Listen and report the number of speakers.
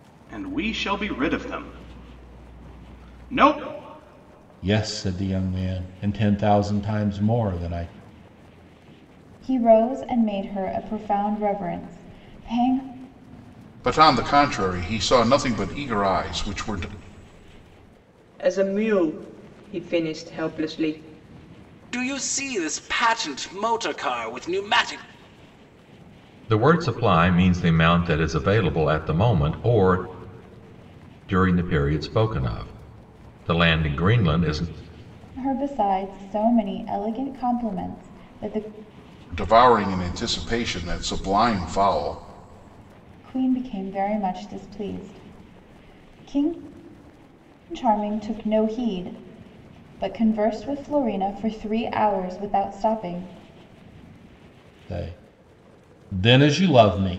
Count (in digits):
7